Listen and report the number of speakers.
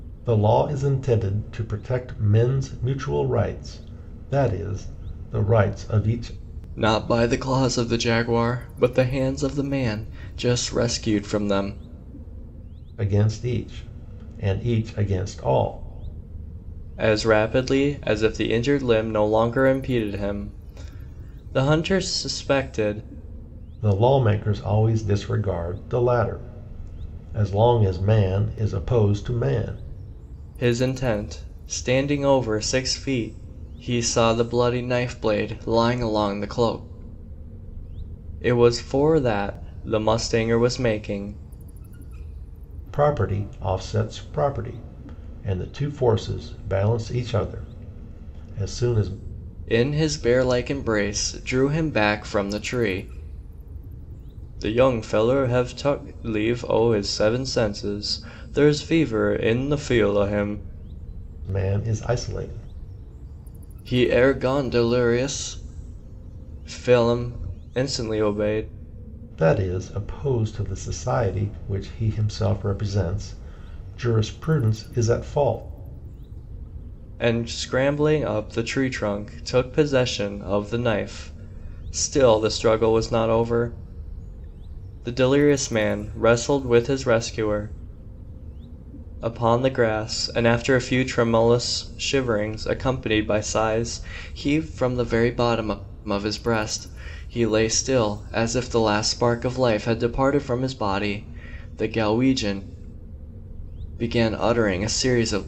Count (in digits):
2